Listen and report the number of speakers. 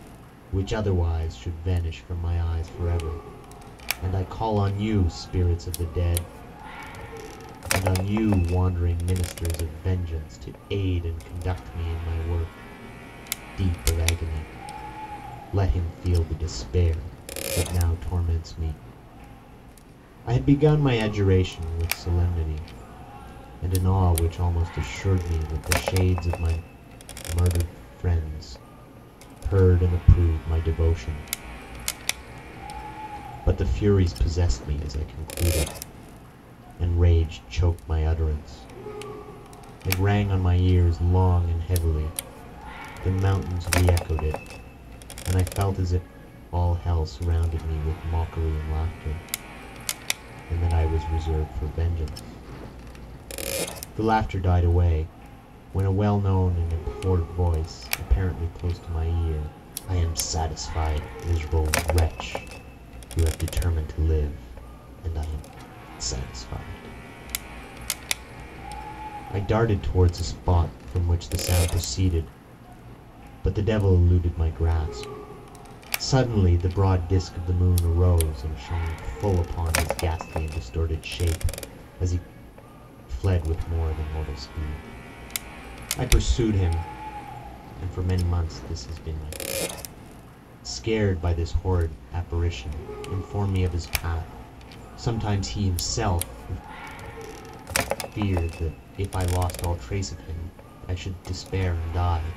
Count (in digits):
1